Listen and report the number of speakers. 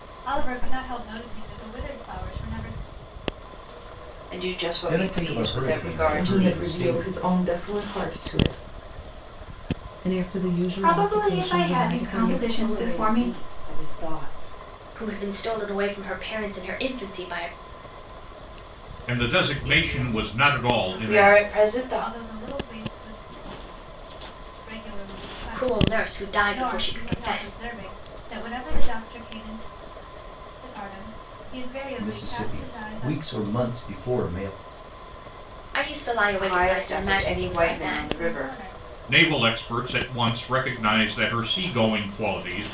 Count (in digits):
9